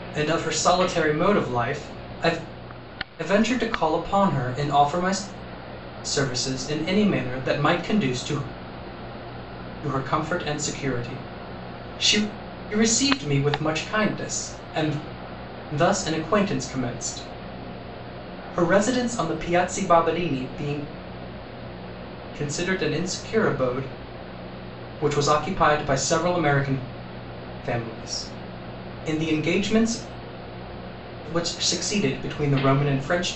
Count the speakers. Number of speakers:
one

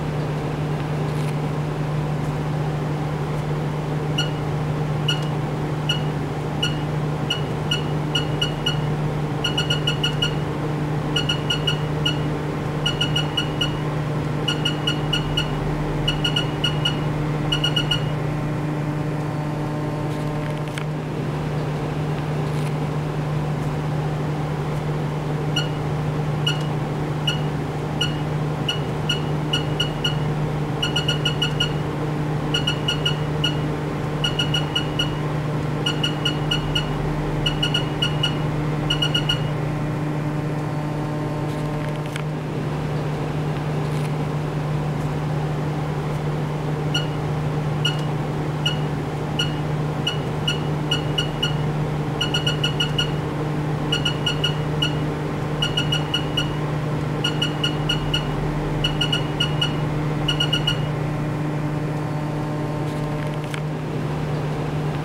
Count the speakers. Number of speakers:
zero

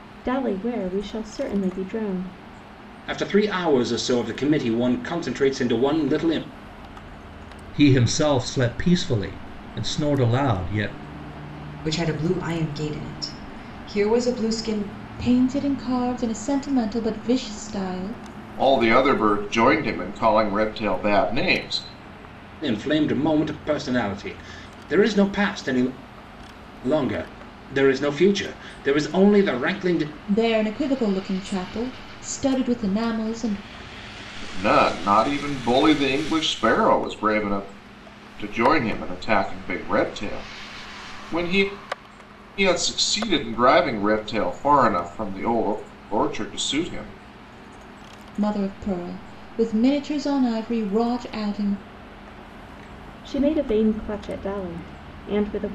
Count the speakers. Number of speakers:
six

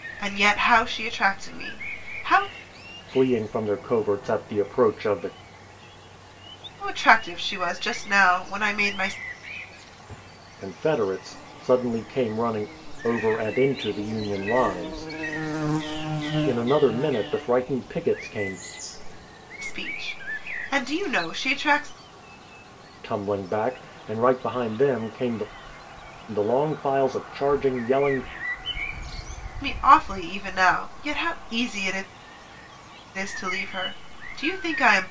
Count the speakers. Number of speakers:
two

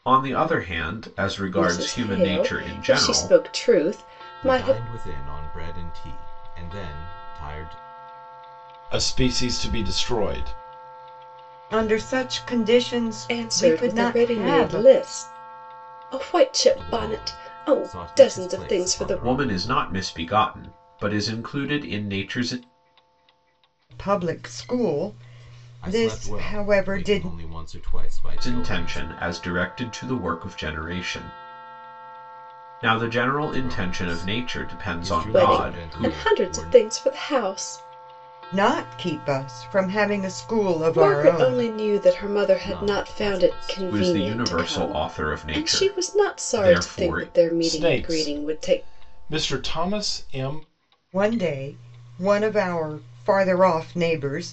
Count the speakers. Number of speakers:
five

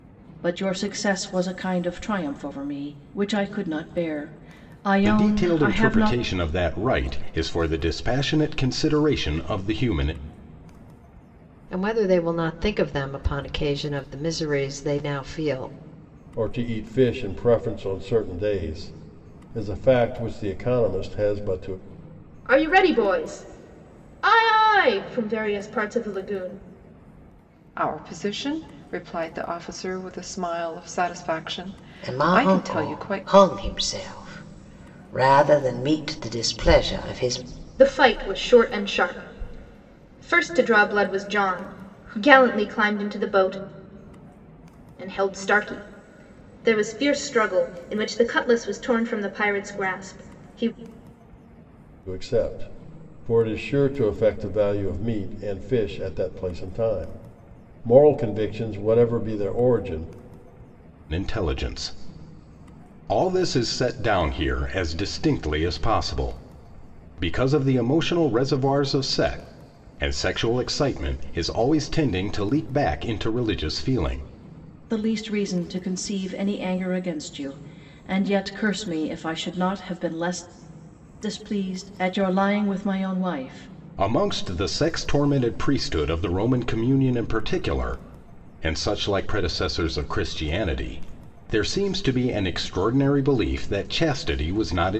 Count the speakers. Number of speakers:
seven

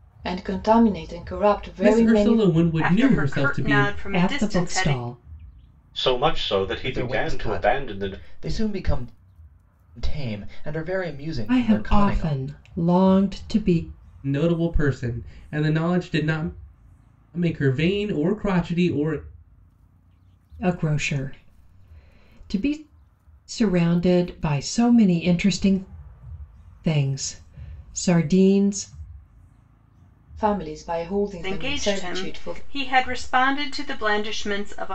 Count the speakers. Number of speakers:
six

